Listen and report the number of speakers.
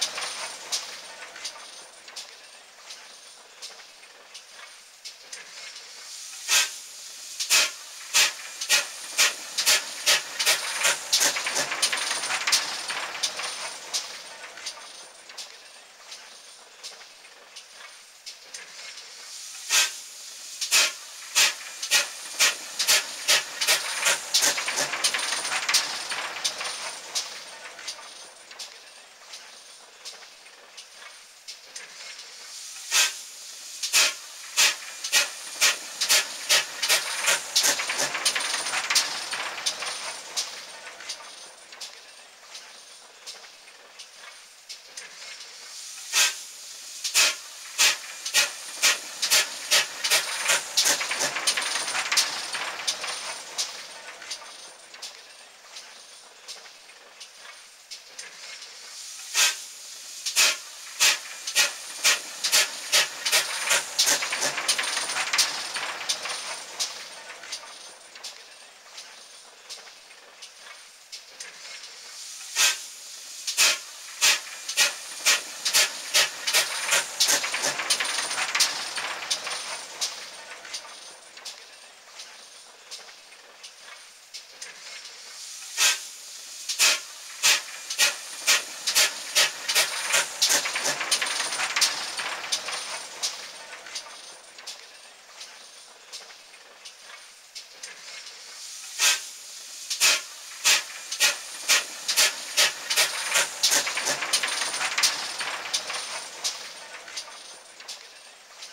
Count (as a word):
zero